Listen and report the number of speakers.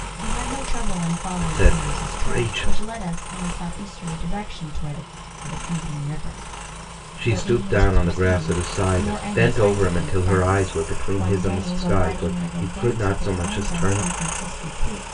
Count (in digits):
2